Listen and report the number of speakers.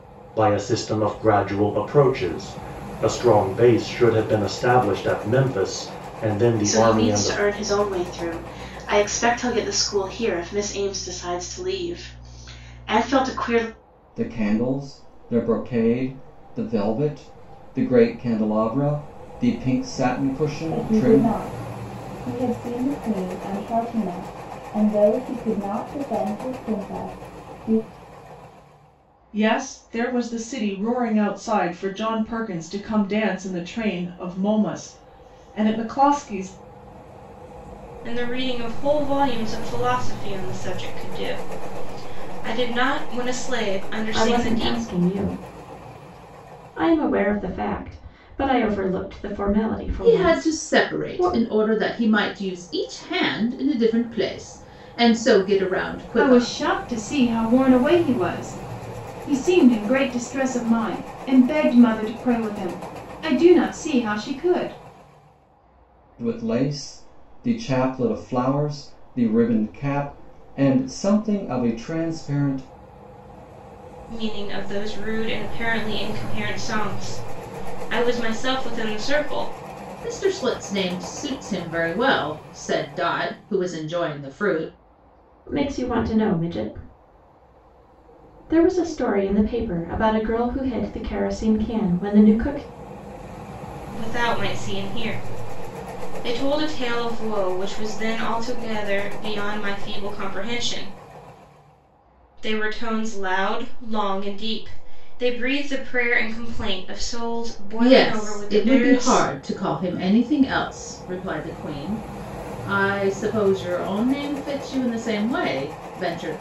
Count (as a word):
nine